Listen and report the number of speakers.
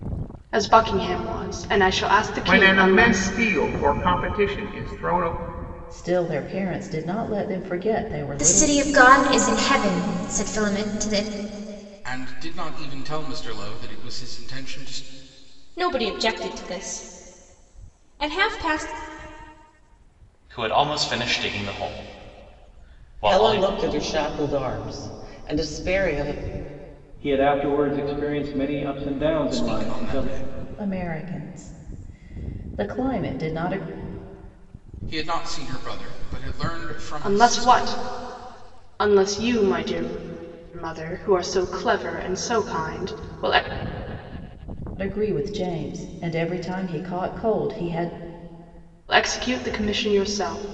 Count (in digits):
9